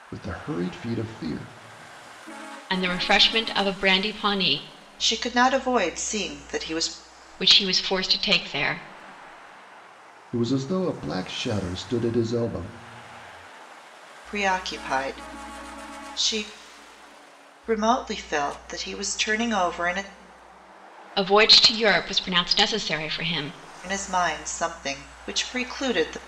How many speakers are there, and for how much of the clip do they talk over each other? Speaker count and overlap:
3, no overlap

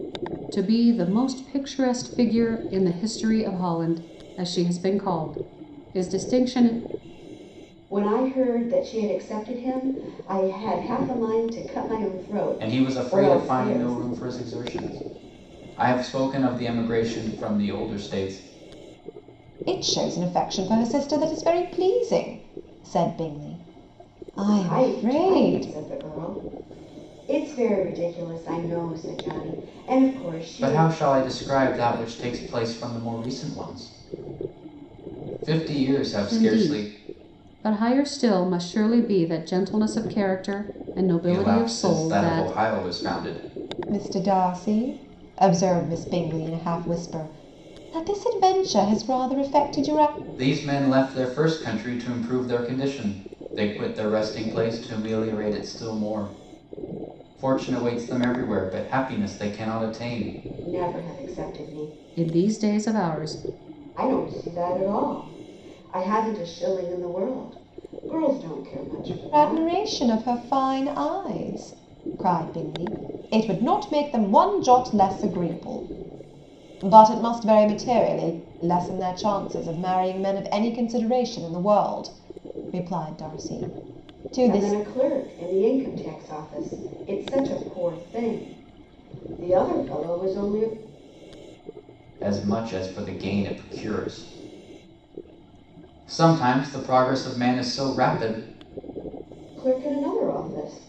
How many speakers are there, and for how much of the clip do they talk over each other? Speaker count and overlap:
4, about 6%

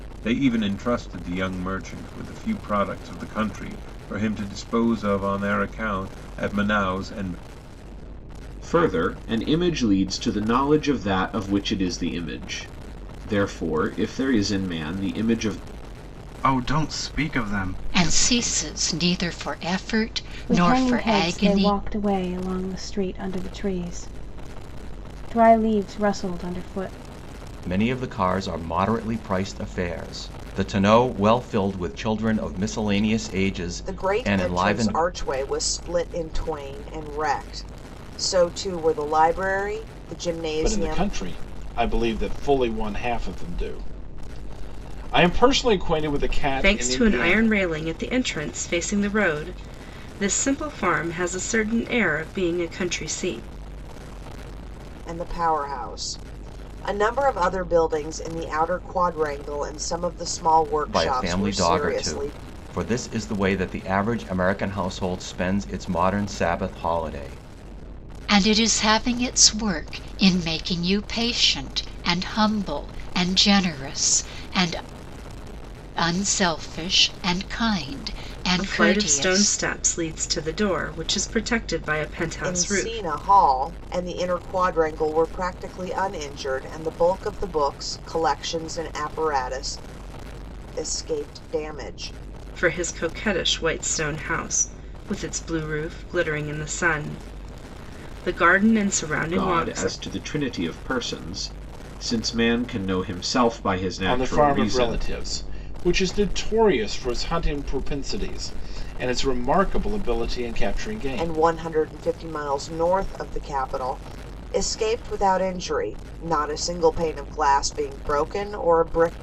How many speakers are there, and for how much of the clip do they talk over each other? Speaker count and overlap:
9, about 8%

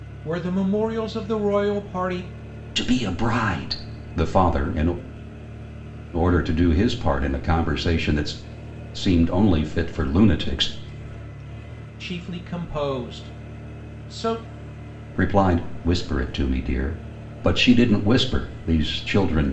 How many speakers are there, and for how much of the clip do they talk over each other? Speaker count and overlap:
2, no overlap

